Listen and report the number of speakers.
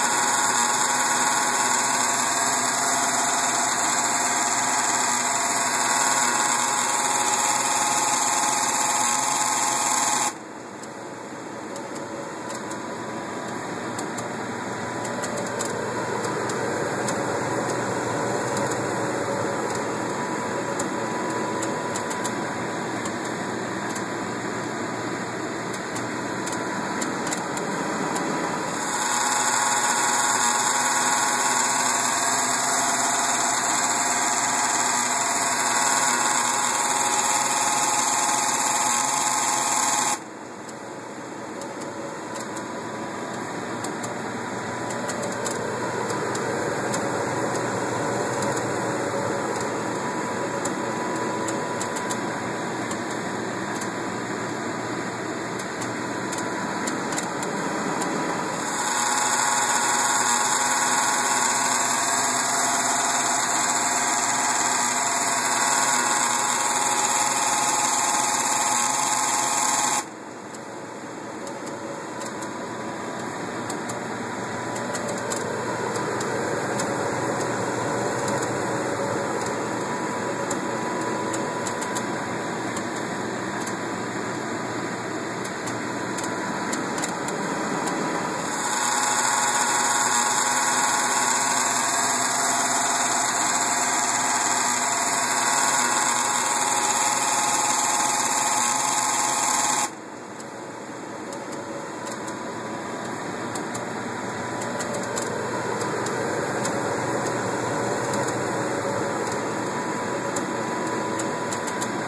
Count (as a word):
zero